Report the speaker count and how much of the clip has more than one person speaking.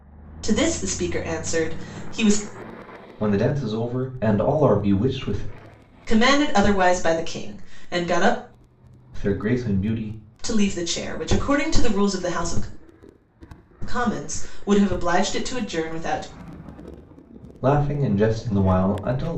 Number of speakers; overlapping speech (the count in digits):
2, no overlap